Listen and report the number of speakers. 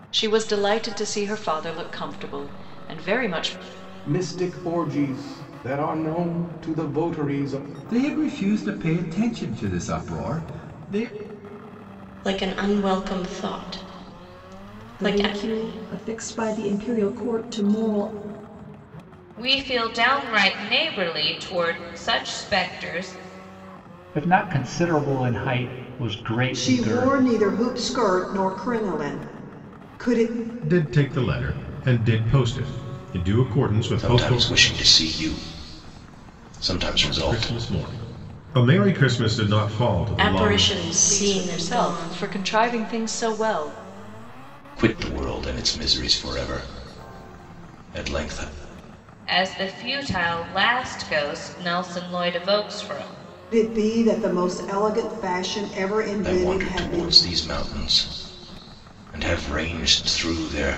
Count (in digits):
10